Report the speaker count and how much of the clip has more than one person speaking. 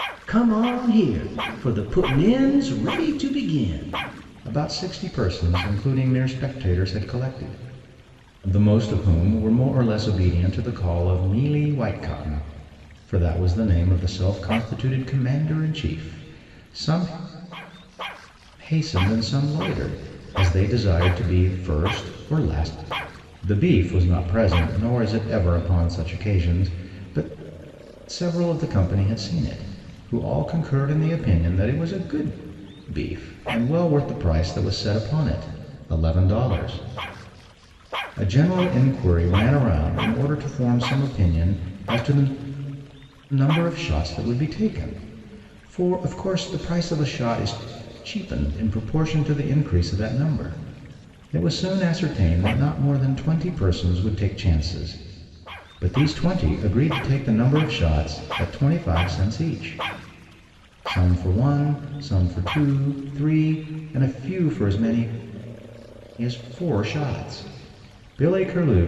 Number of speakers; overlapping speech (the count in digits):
1, no overlap